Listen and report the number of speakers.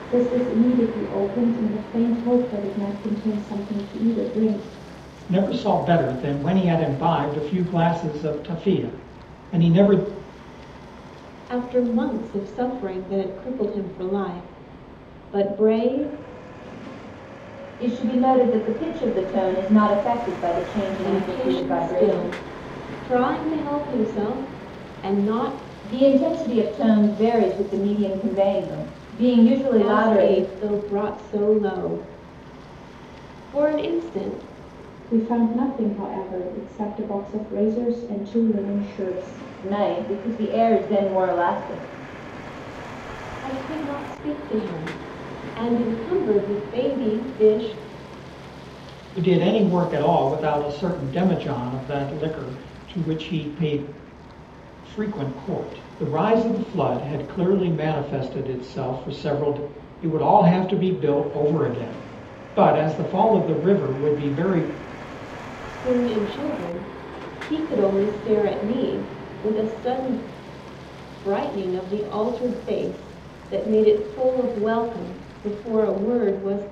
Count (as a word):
four